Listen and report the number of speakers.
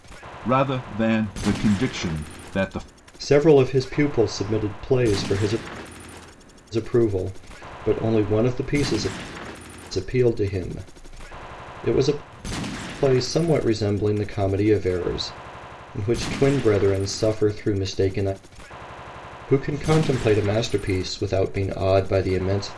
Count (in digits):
2